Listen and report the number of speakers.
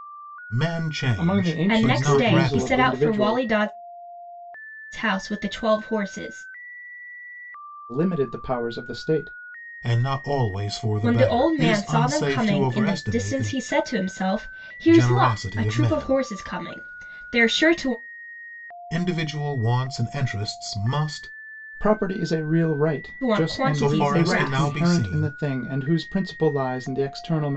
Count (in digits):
3